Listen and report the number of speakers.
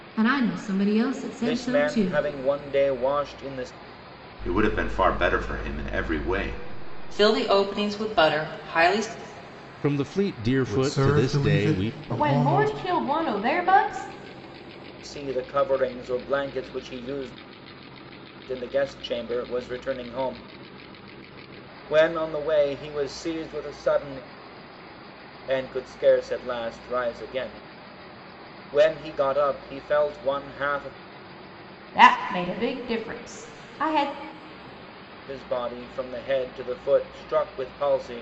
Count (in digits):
7